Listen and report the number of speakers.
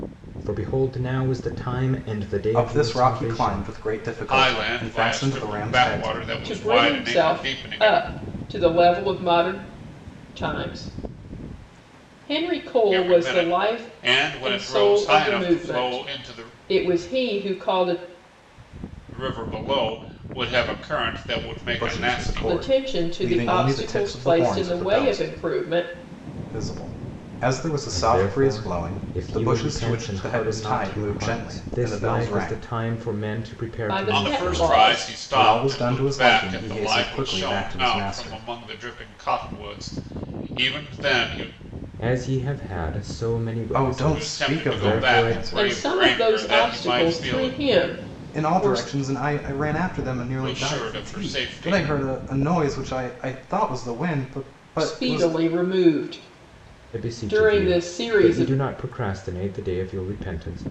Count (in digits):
4